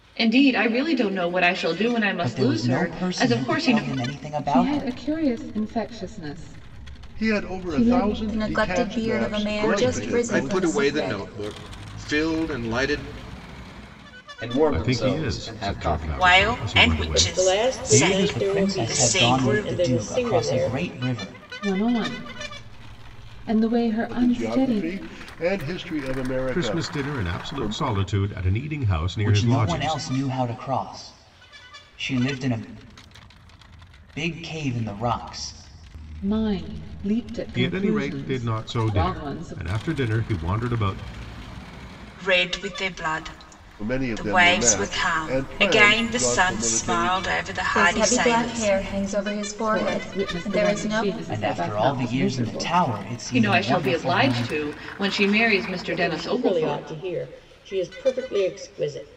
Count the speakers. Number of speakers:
ten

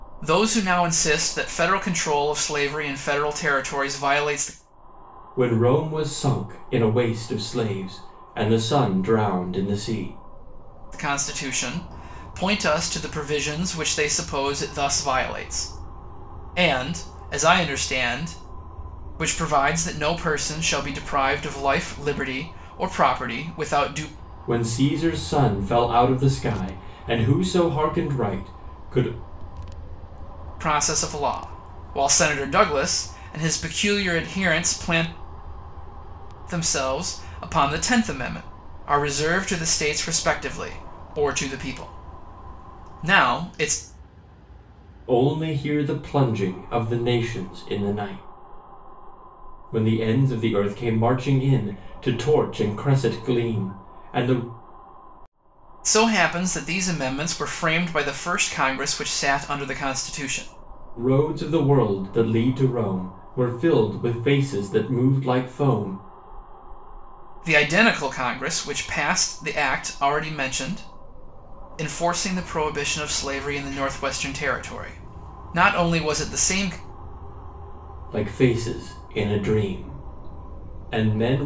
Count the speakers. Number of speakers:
two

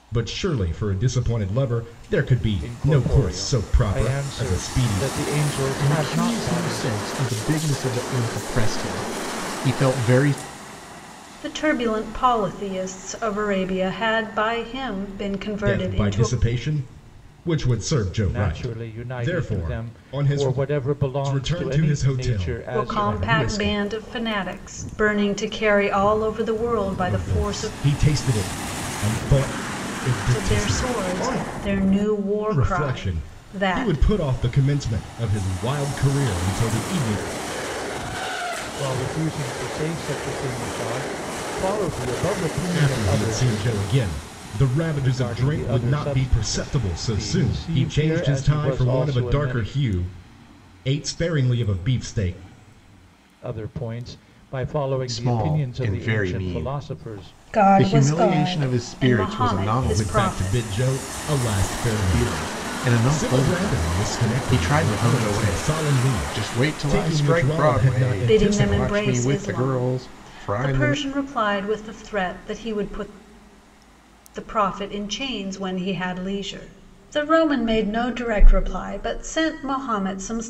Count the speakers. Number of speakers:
four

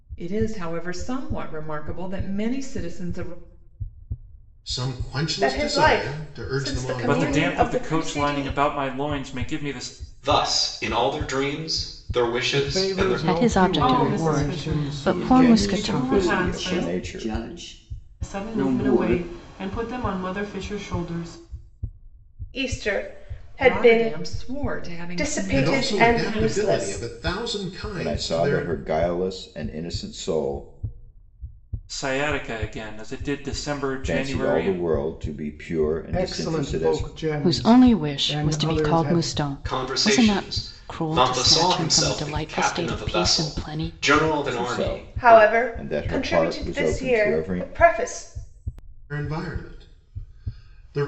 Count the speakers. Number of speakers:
ten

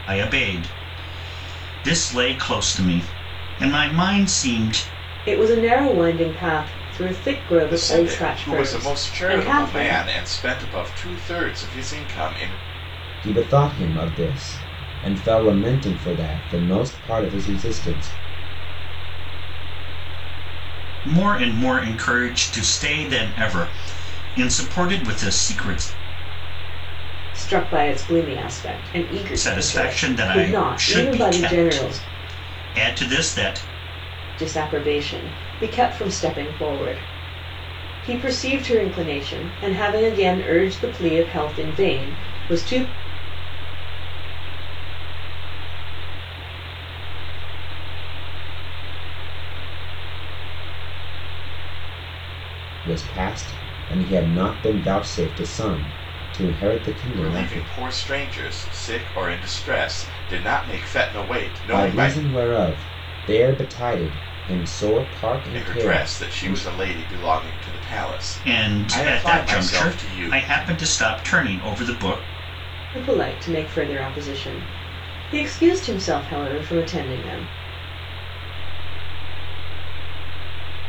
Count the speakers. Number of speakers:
five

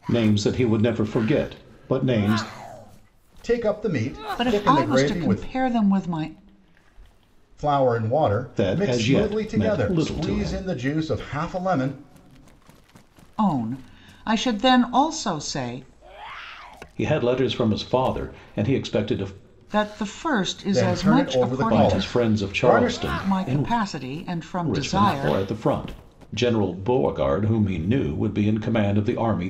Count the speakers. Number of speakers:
three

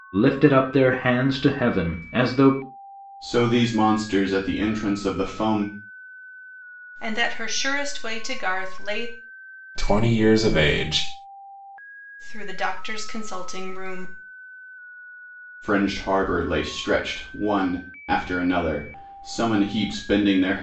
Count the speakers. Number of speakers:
four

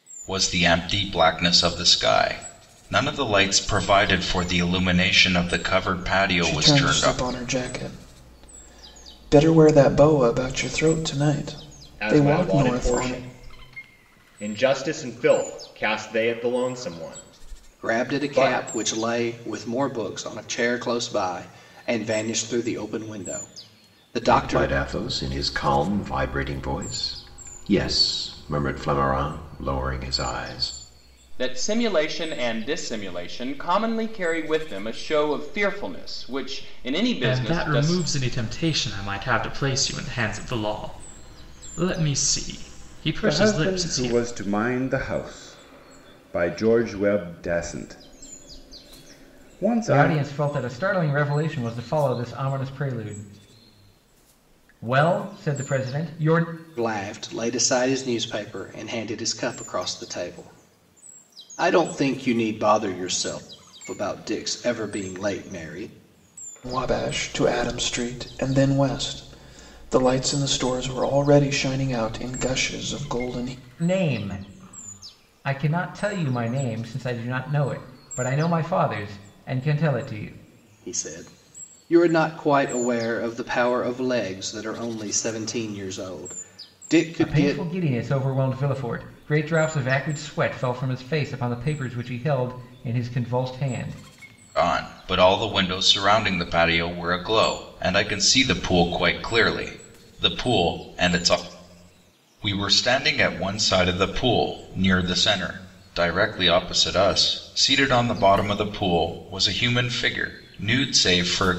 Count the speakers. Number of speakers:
nine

